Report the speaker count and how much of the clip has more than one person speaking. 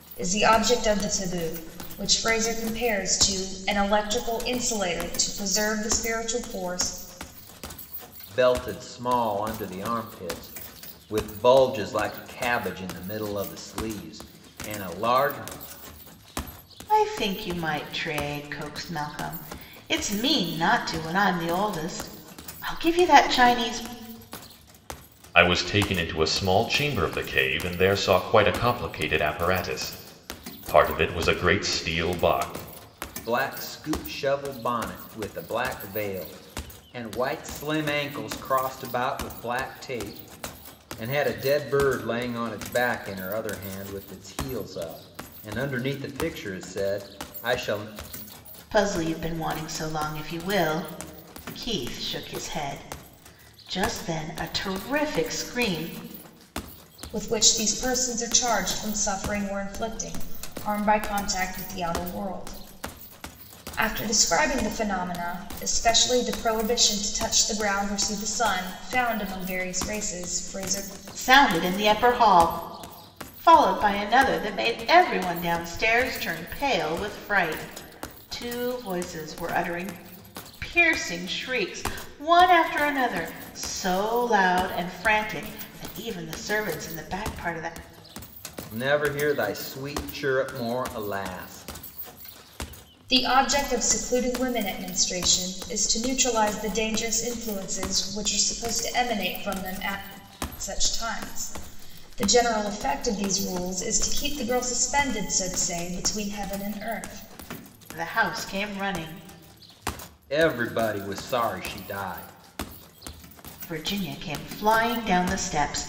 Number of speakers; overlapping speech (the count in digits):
4, no overlap